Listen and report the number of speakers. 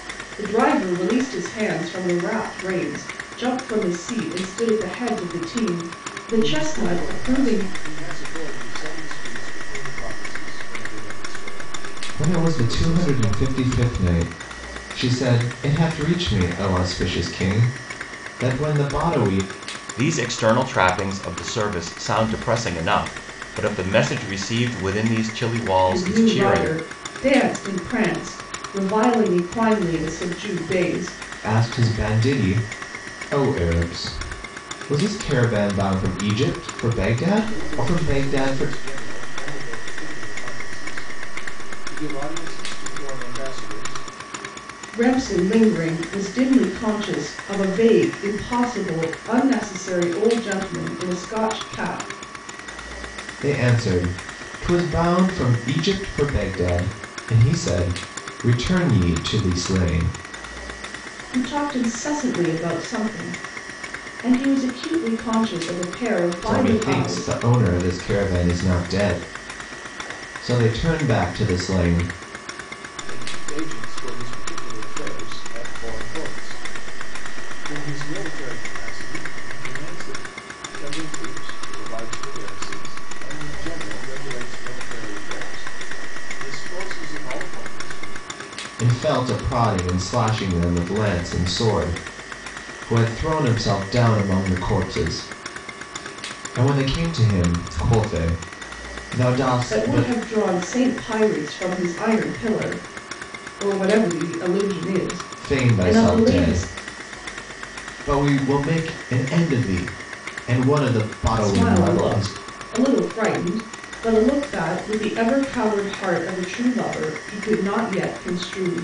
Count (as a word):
four